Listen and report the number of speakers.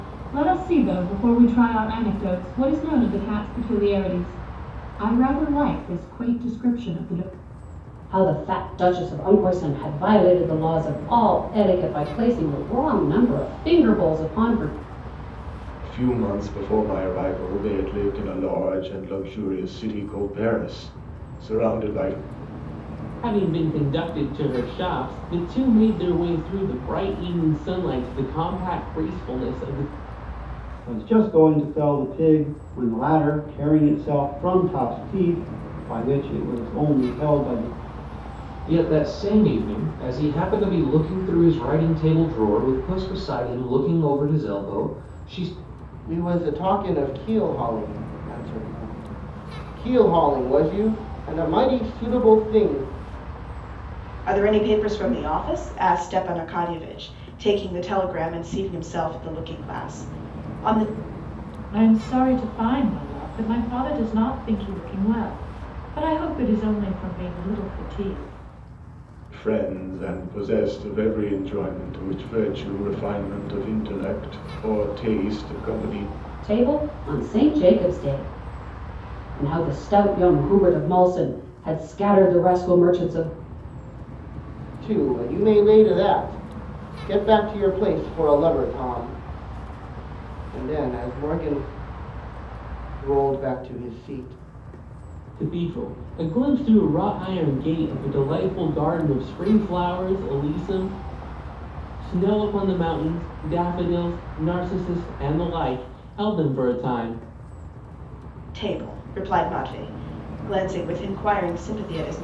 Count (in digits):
9